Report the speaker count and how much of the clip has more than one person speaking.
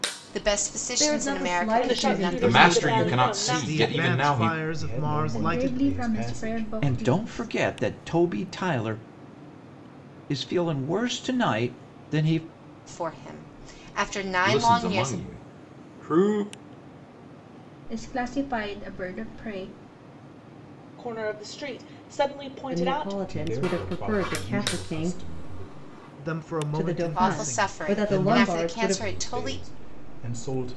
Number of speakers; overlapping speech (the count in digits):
8, about 41%